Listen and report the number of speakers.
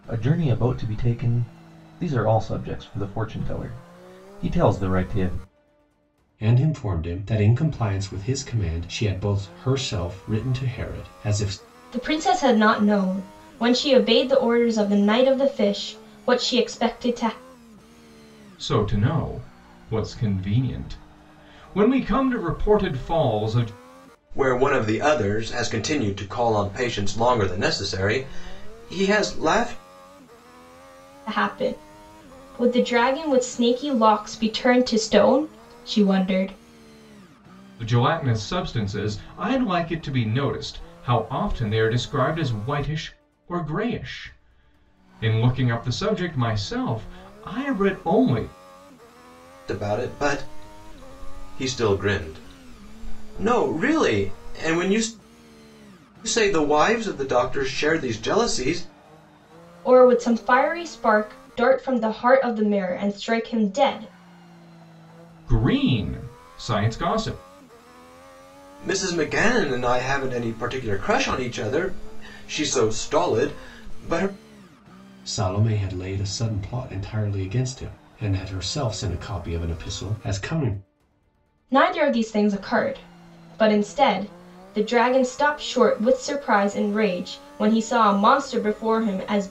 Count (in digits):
5